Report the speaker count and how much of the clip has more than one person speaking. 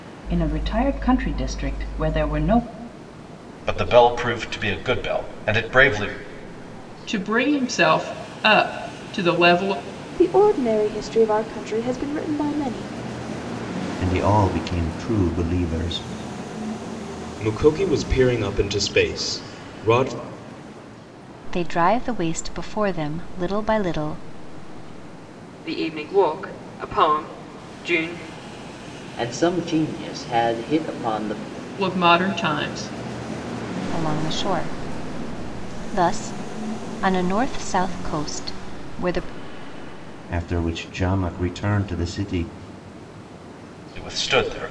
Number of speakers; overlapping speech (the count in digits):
9, no overlap